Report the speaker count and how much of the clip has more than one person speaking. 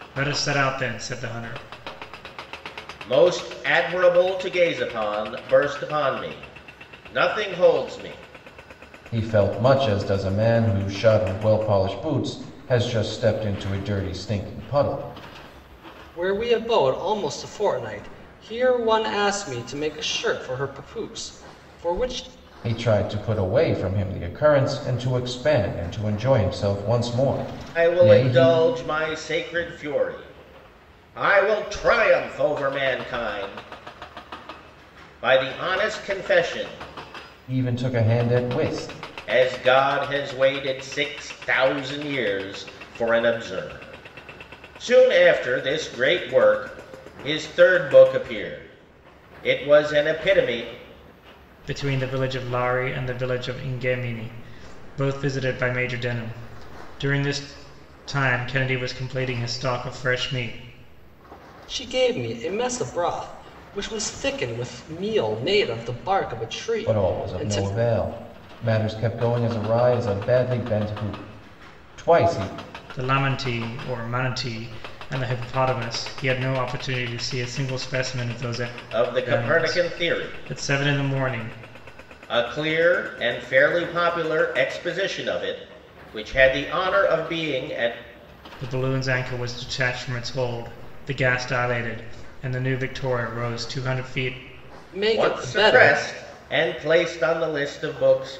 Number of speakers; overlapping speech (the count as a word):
four, about 4%